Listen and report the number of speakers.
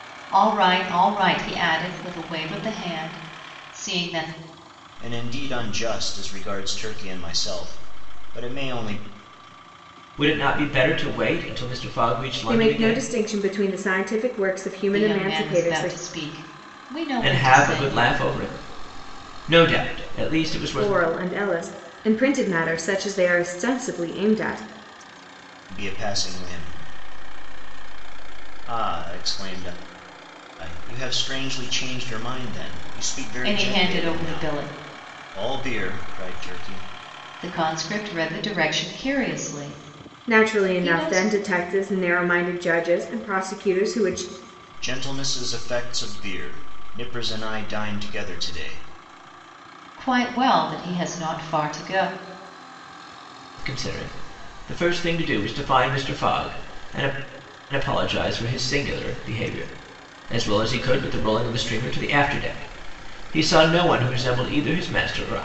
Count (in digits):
4